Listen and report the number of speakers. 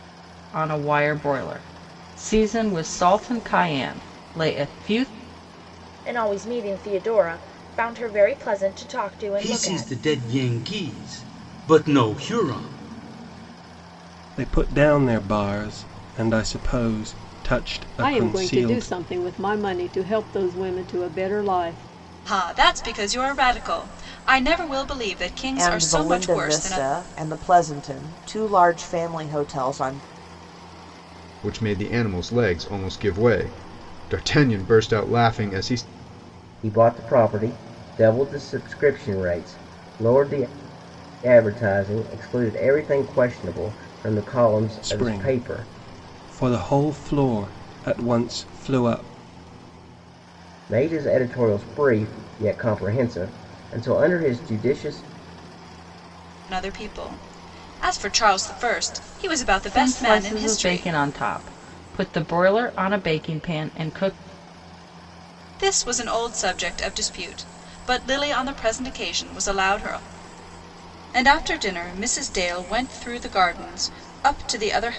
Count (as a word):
nine